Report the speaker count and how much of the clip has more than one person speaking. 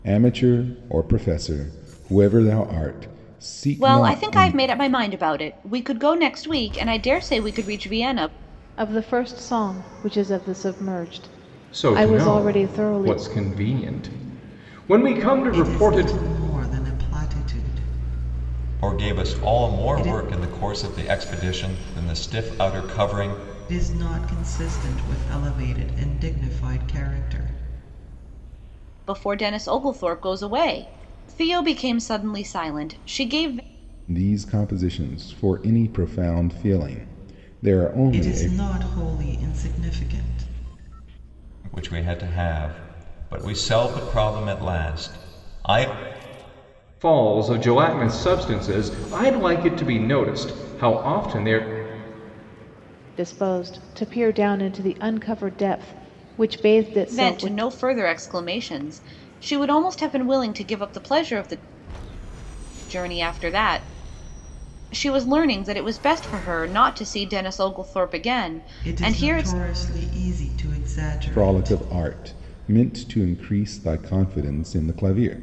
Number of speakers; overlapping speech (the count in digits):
6, about 9%